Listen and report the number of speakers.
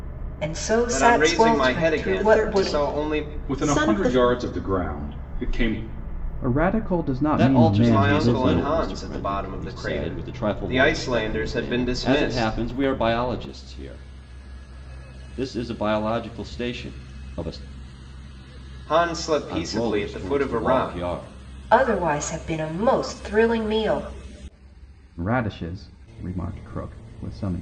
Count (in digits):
6